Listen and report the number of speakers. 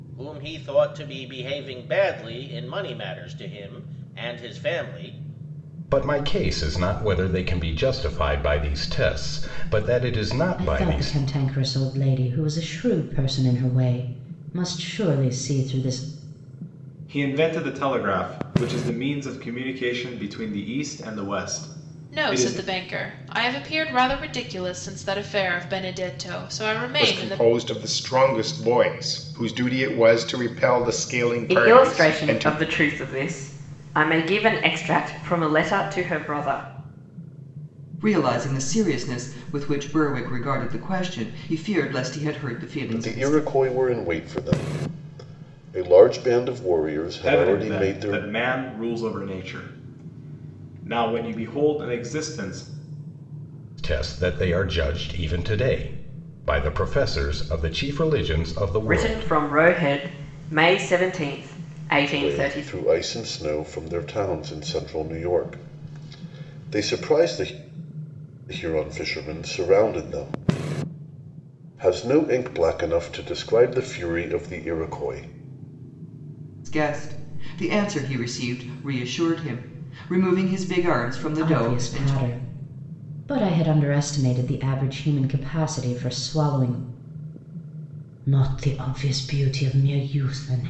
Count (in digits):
9